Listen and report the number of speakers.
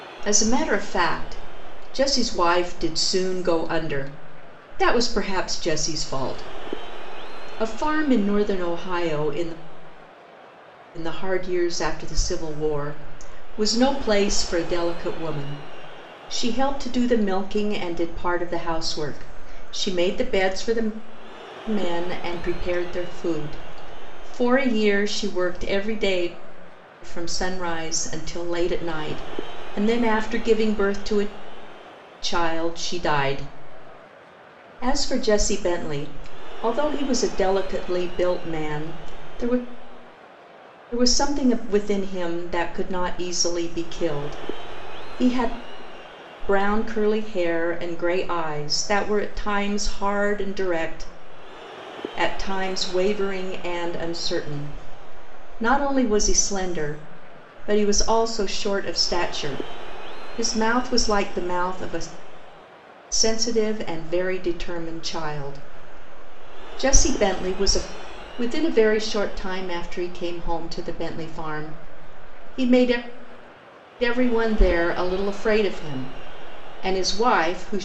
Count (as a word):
one